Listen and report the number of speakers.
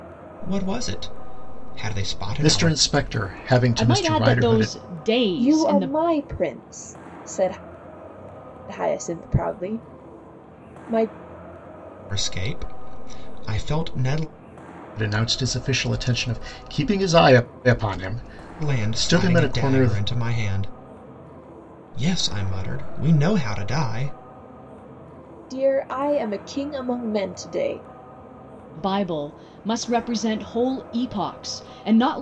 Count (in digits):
4